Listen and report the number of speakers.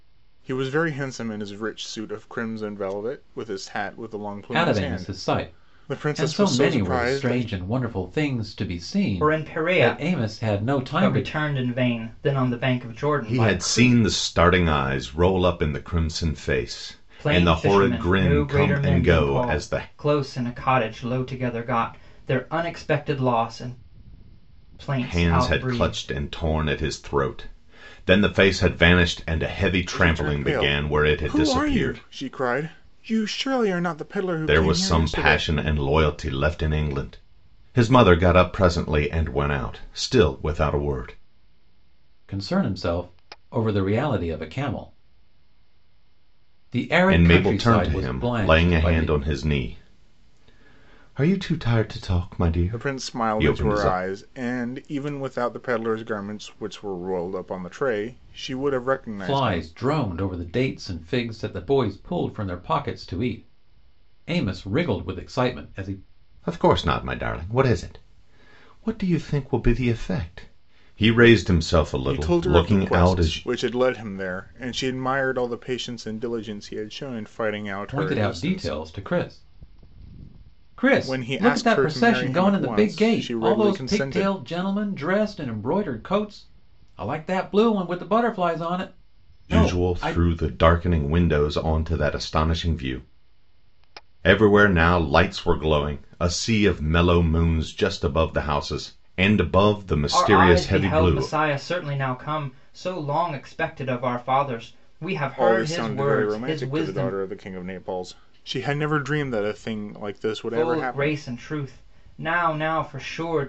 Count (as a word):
four